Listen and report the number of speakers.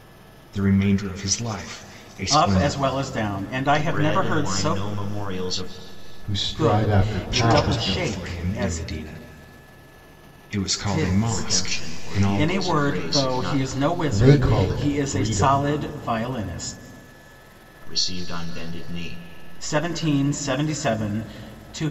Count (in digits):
4